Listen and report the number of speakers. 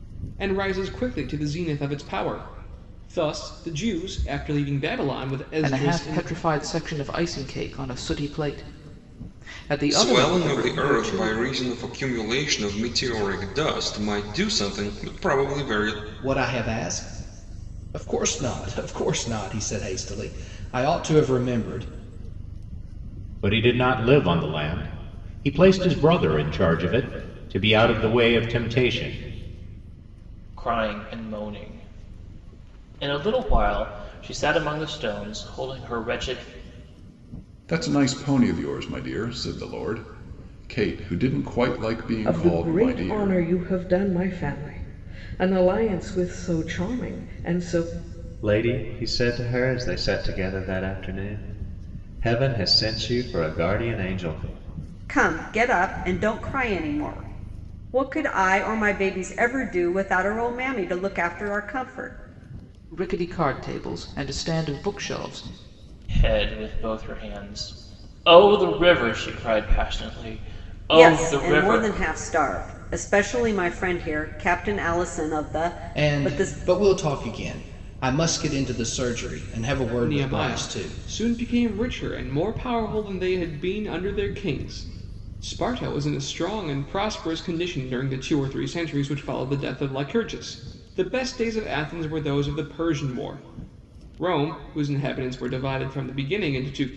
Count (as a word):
ten